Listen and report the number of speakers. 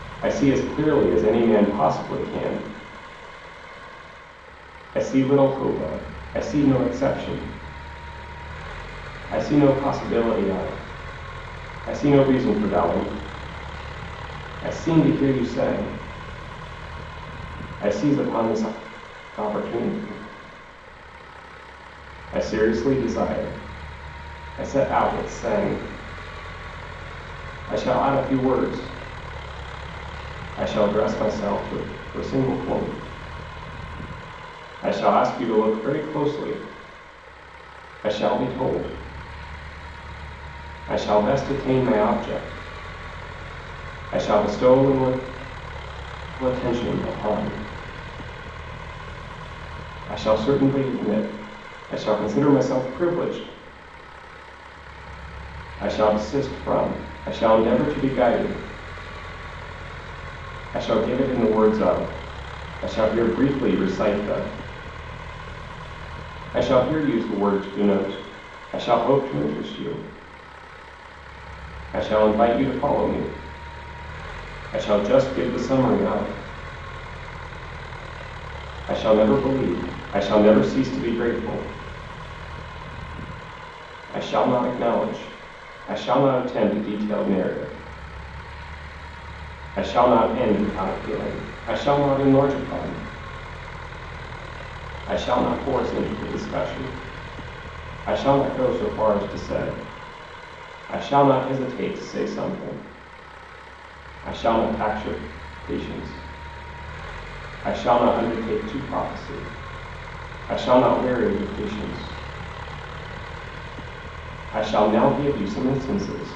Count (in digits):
1